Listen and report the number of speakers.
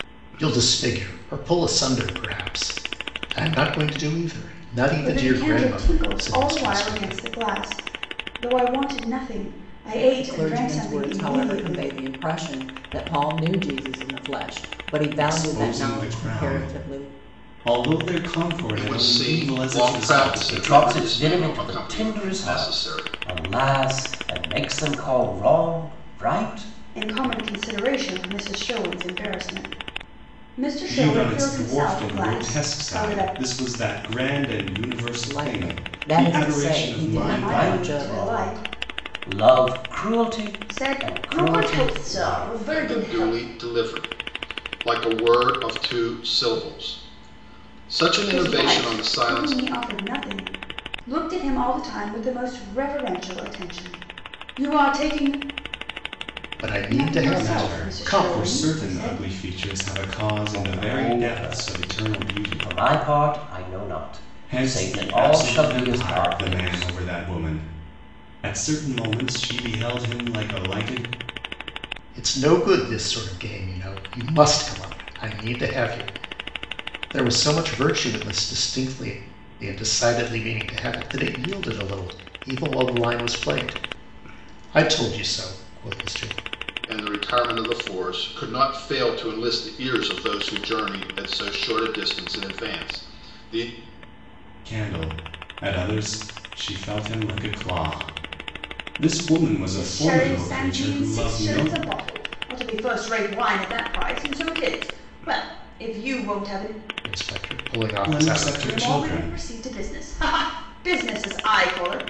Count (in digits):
6